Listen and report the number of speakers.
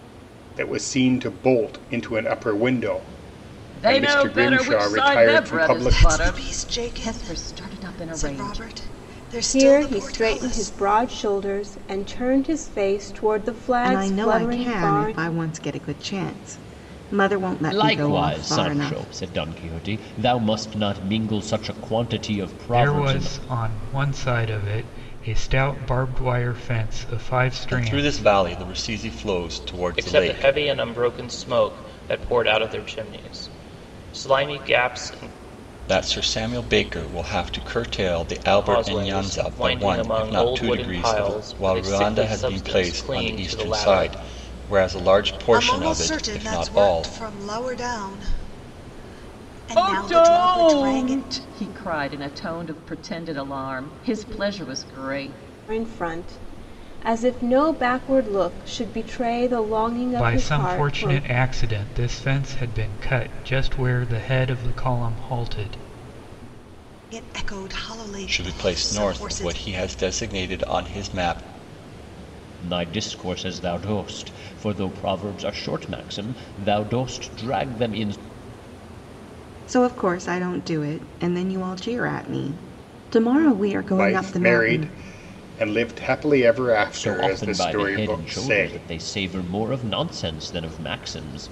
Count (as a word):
nine